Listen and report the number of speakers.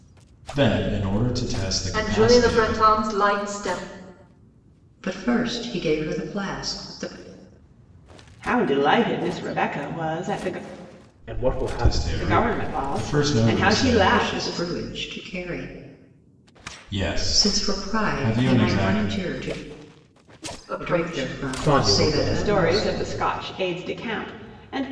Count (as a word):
five